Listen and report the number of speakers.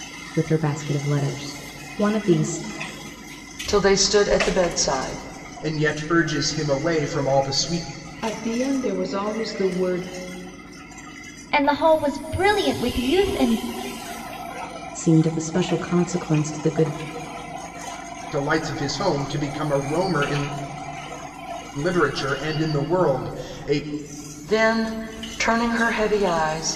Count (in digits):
5